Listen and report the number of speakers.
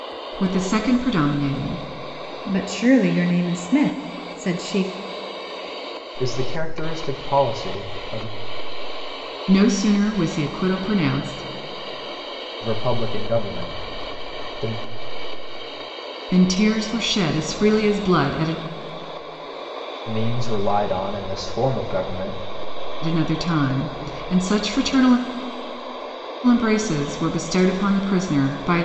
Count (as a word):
three